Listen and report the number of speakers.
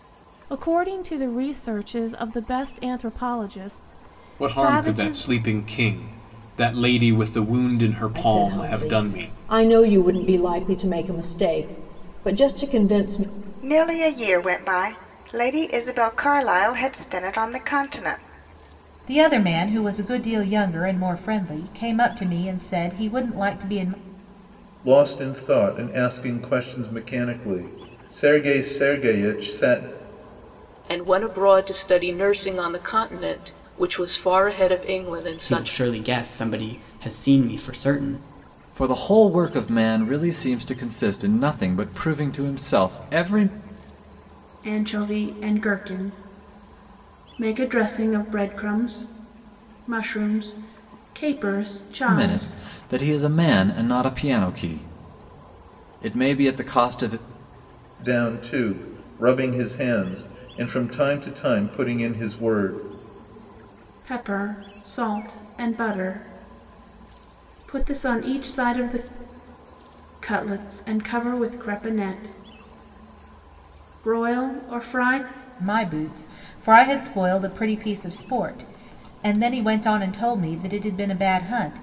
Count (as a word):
ten